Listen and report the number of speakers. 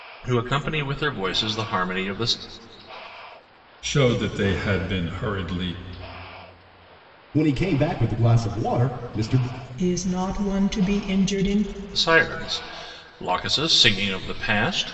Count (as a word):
four